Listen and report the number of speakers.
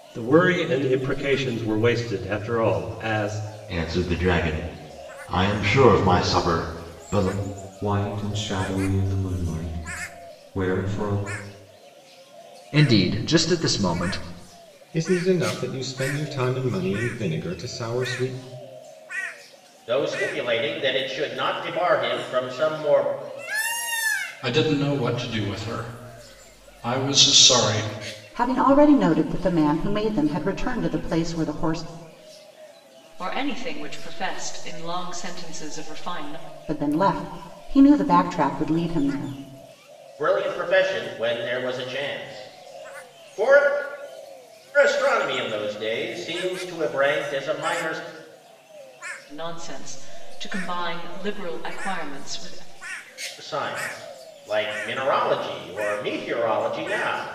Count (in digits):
9